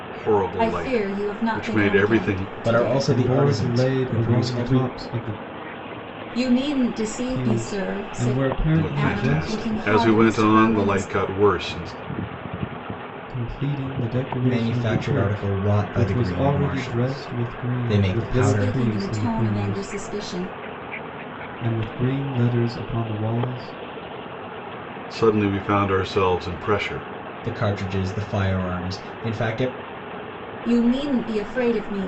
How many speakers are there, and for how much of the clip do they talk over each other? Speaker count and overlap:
4, about 40%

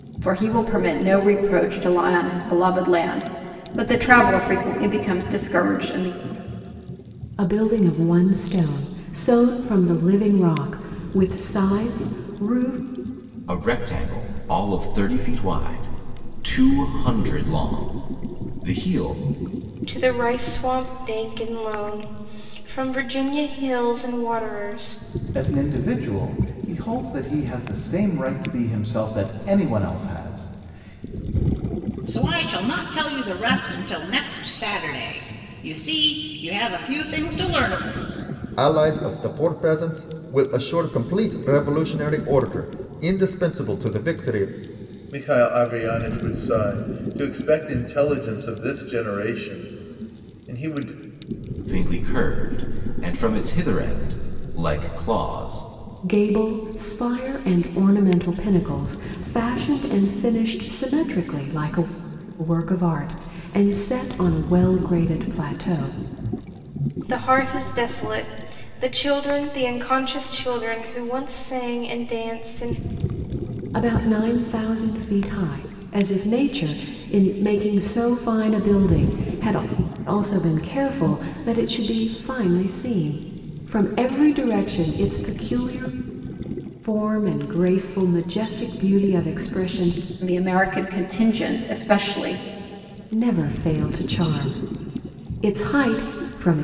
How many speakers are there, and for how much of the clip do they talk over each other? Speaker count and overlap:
8, no overlap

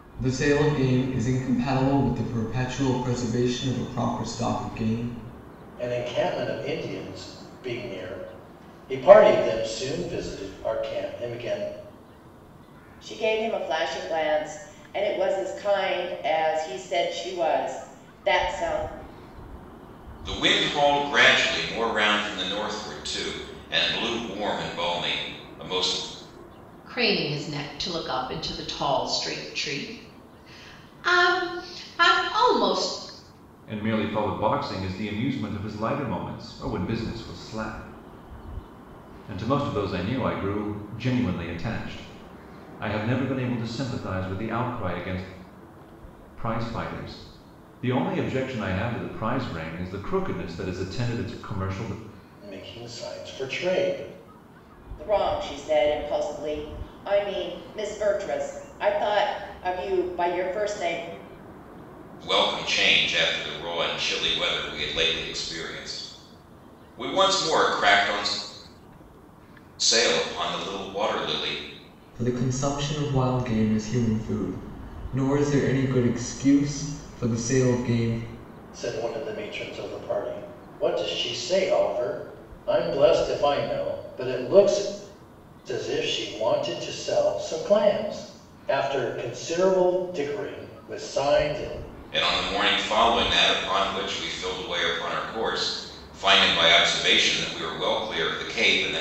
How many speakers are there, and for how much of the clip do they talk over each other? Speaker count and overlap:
6, no overlap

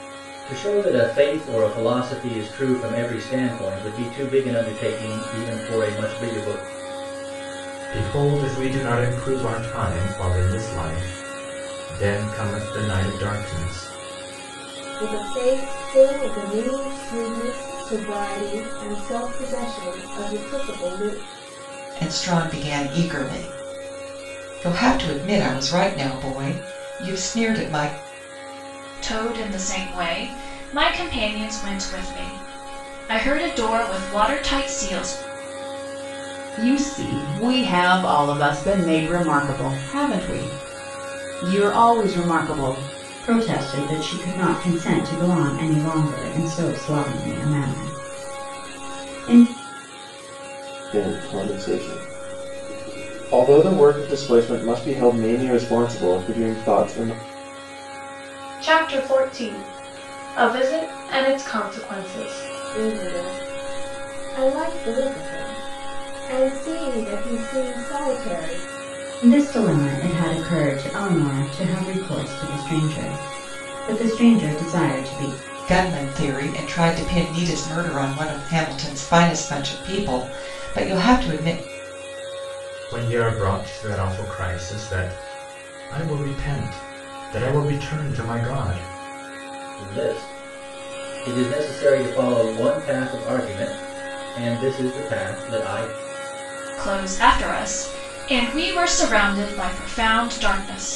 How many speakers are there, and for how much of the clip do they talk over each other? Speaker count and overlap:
9, no overlap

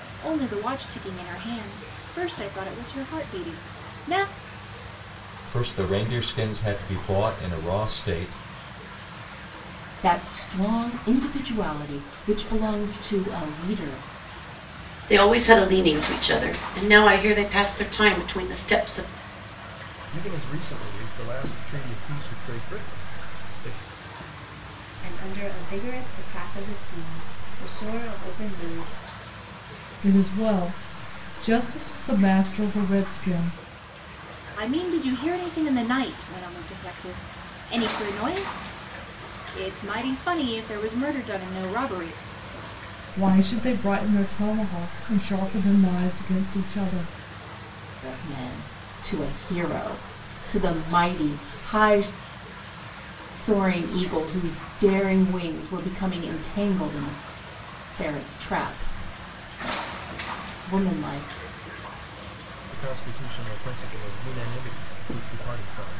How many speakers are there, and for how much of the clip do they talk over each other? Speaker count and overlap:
7, no overlap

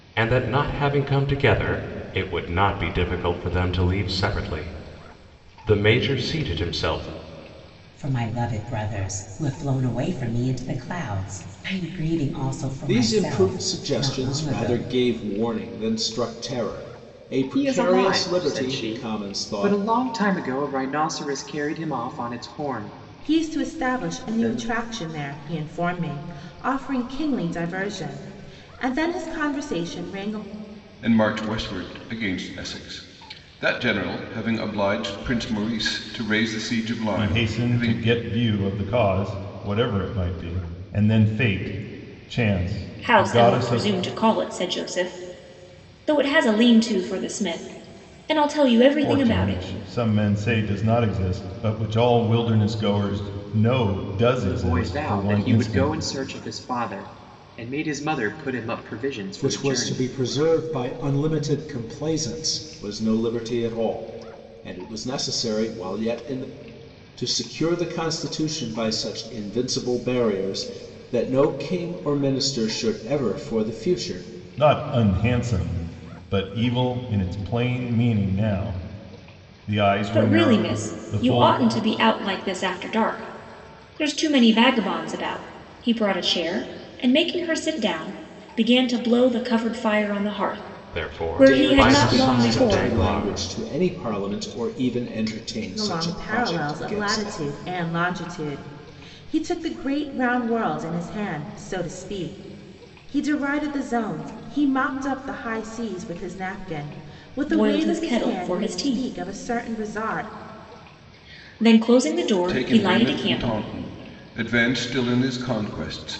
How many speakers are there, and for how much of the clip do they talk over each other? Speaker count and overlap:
8, about 18%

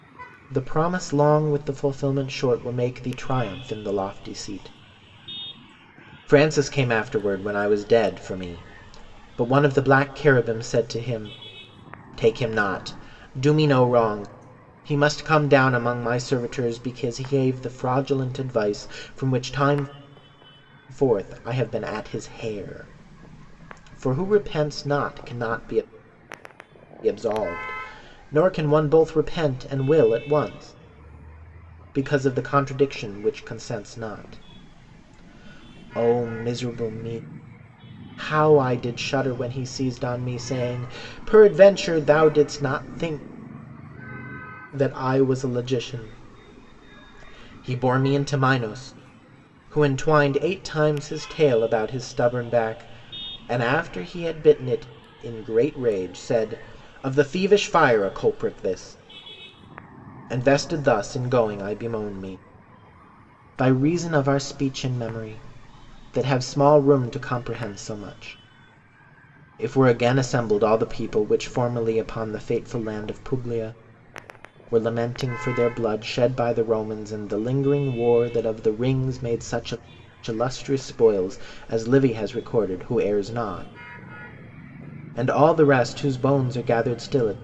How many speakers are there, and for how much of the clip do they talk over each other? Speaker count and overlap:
1, no overlap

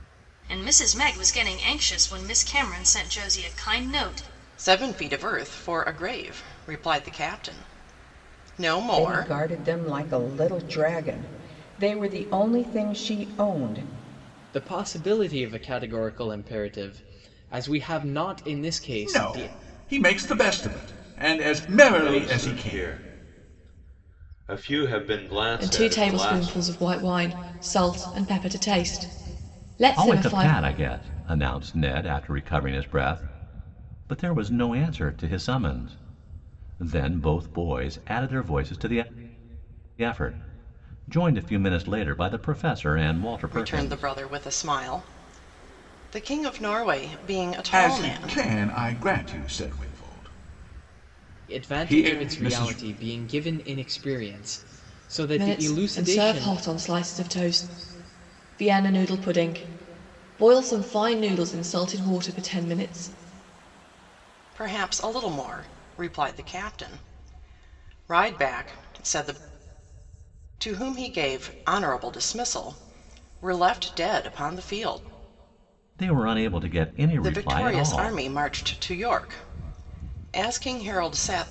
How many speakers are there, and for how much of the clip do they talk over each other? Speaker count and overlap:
8, about 11%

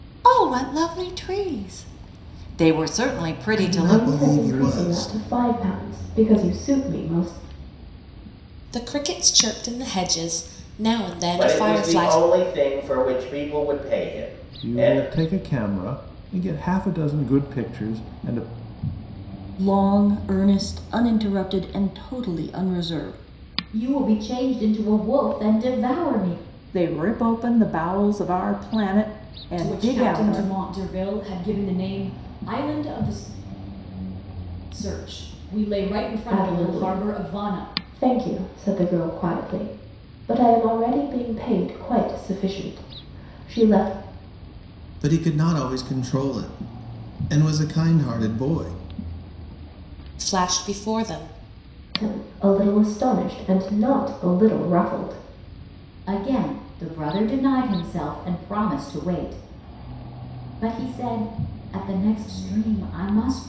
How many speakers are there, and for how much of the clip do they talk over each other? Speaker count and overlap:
10, about 8%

